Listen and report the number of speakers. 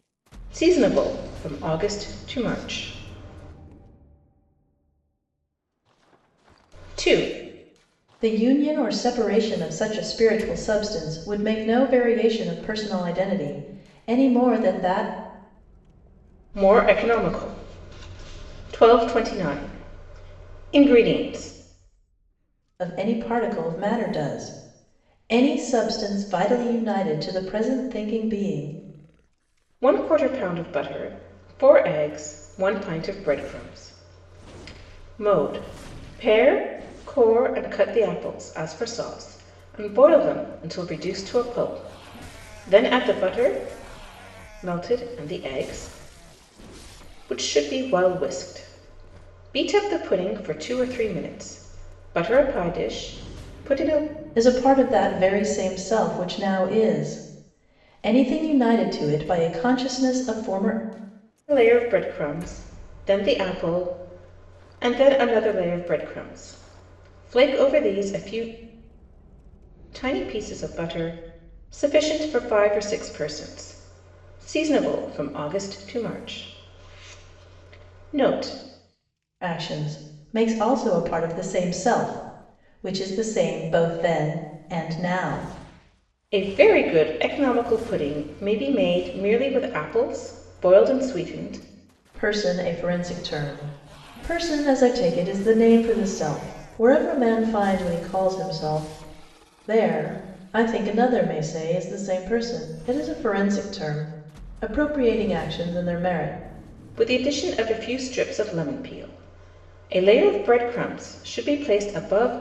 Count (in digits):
2